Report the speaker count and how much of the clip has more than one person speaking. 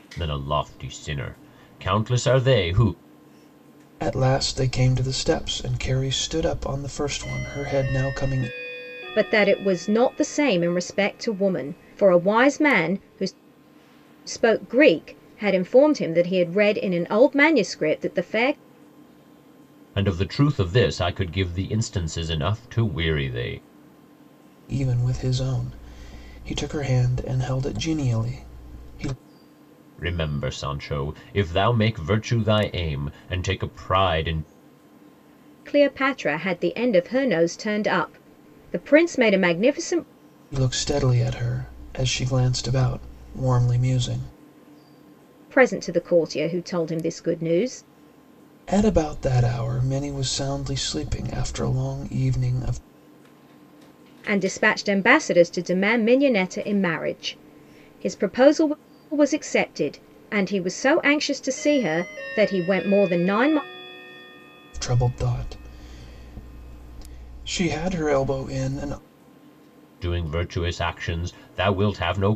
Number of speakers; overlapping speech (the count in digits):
3, no overlap